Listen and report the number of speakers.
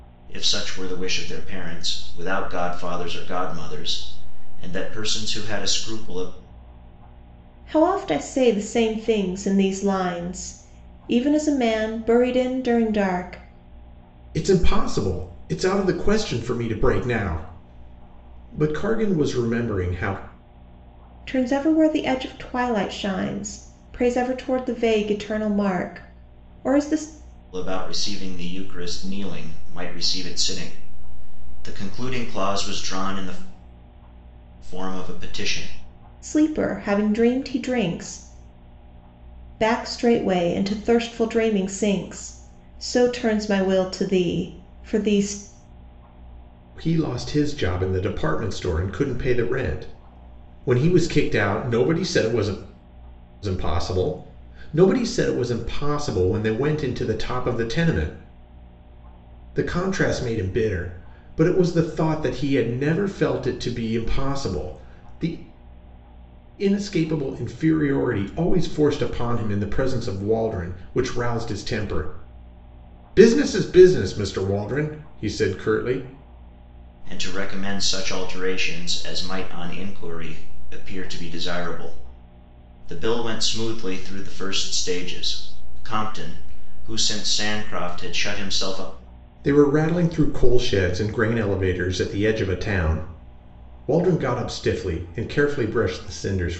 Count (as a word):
three